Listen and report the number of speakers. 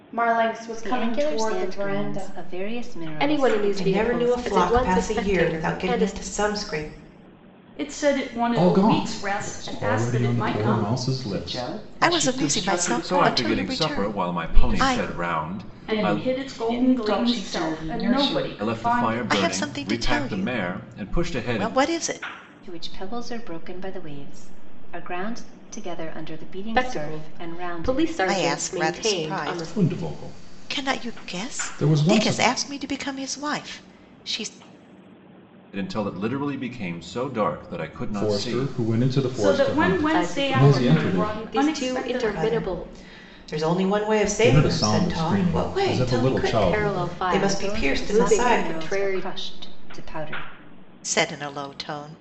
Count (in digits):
9